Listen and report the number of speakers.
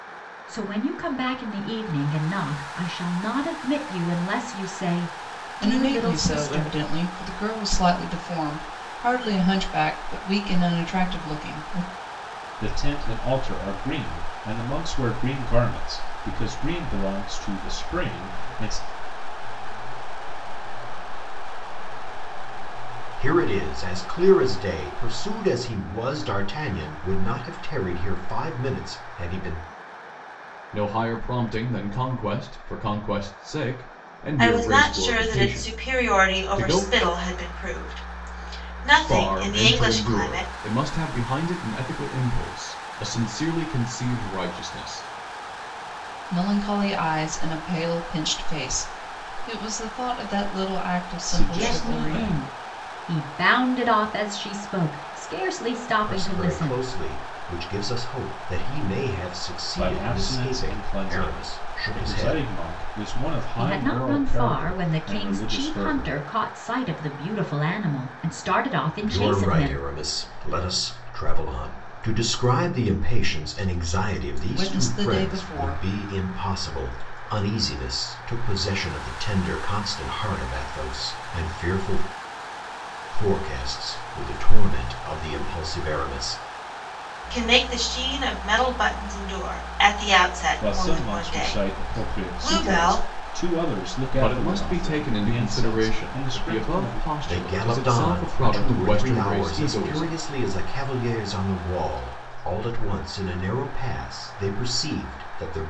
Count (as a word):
seven